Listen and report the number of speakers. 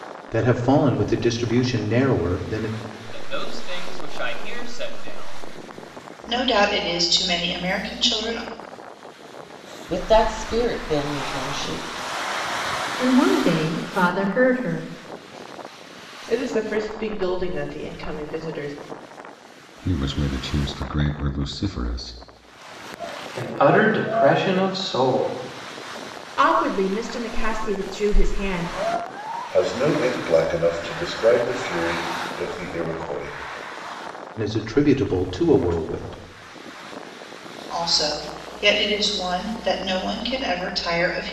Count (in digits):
10